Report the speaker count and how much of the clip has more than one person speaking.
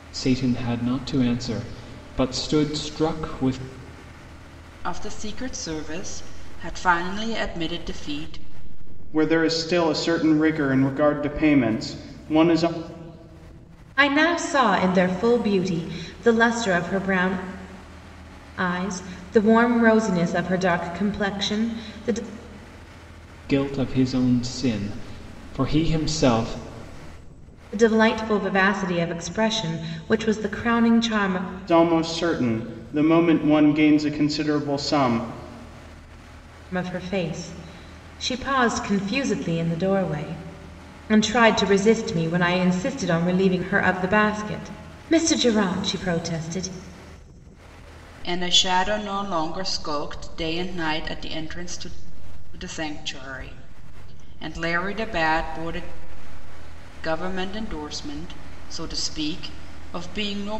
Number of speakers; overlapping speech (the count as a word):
four, no overlap